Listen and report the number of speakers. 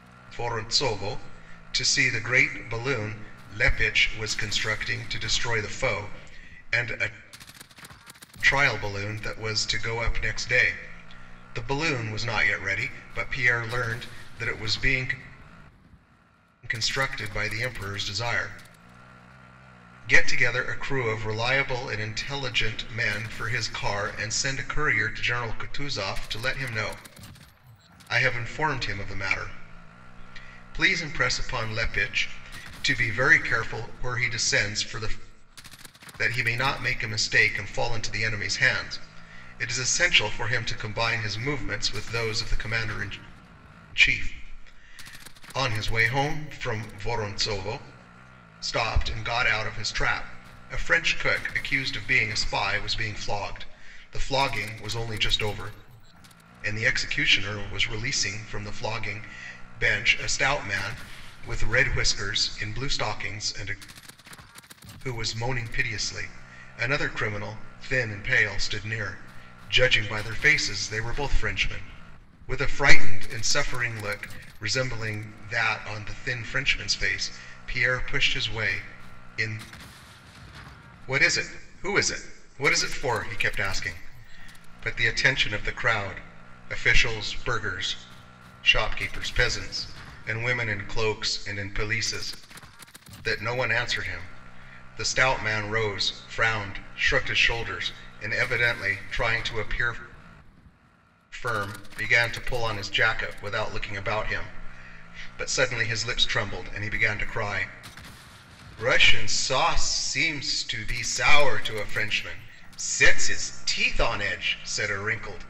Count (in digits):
1